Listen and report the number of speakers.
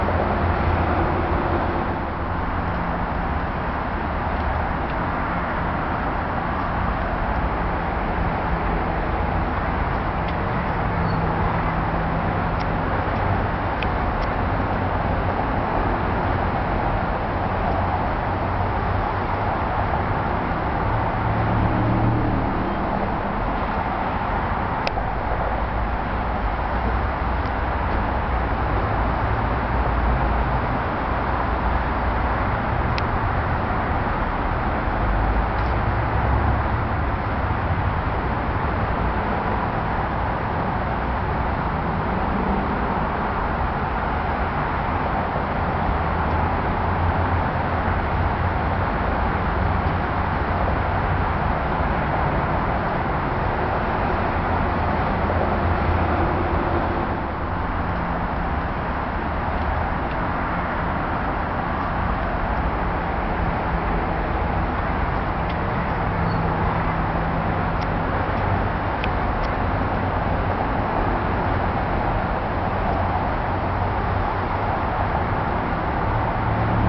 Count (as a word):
zero